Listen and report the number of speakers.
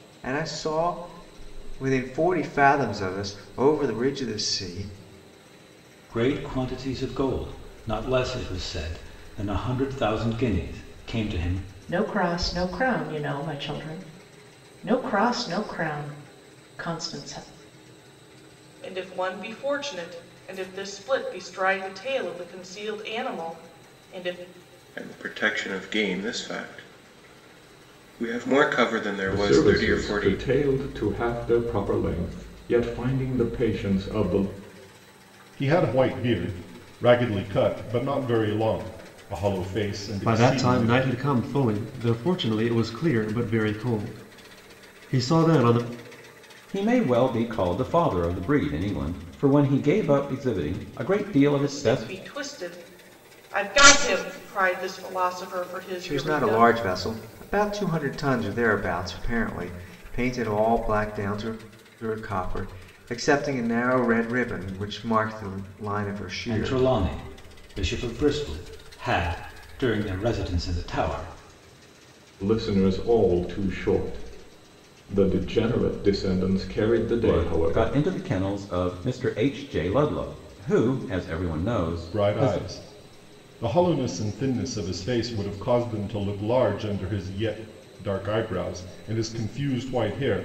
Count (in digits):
9